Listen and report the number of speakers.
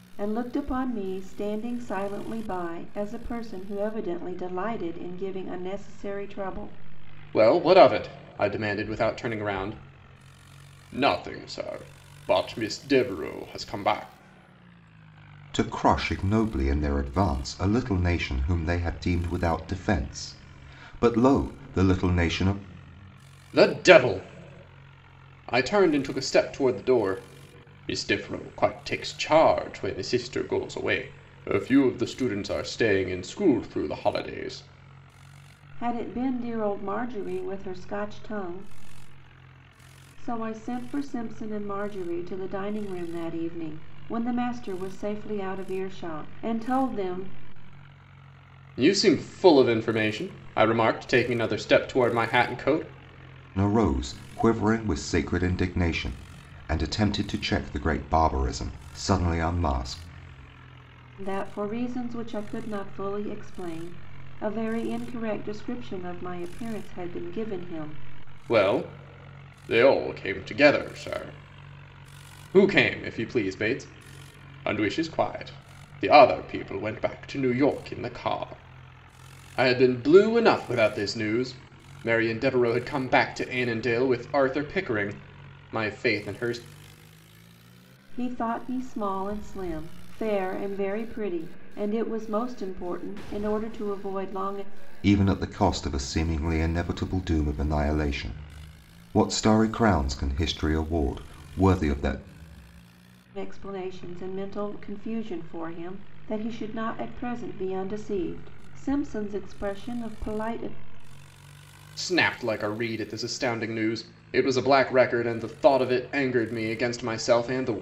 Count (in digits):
3